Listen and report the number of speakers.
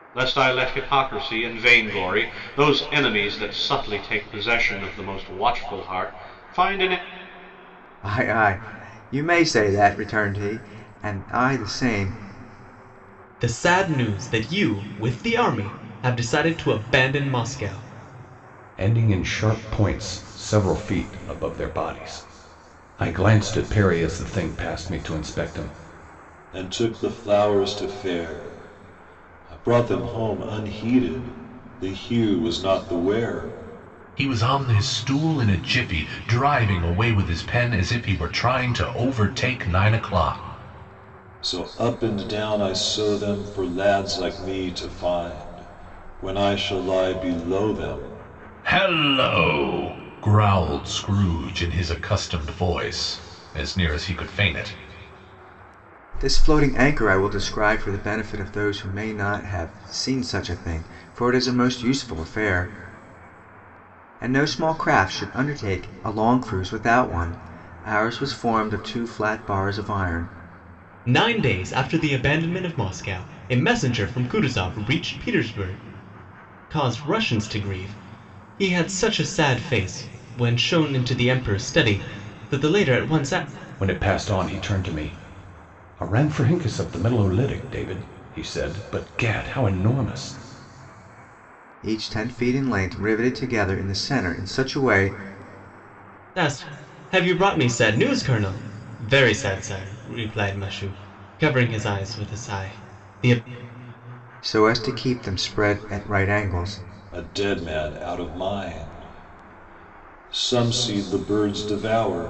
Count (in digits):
6